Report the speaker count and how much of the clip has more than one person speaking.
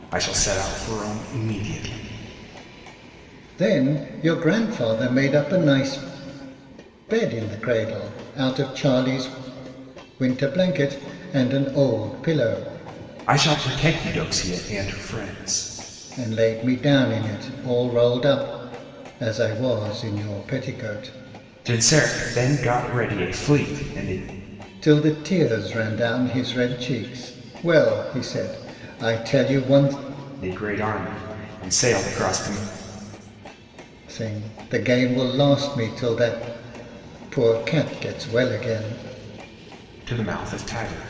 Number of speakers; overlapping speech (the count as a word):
two, no overlap